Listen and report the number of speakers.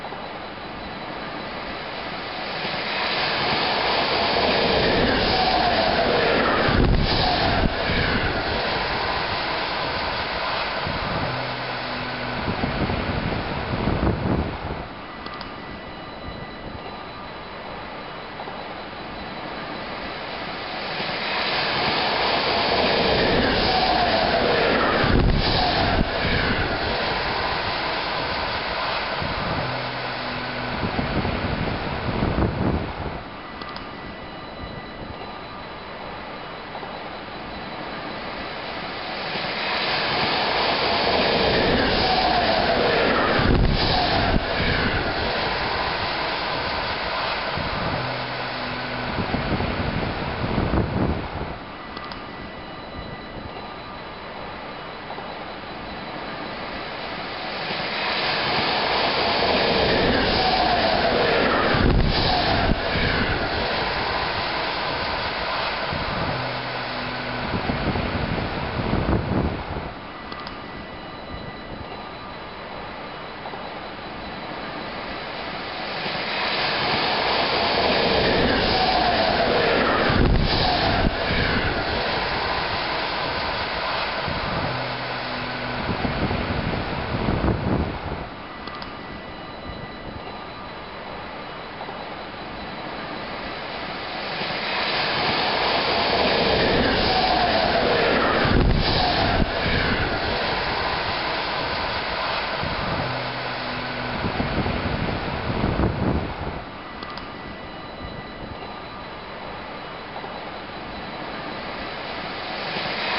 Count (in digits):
0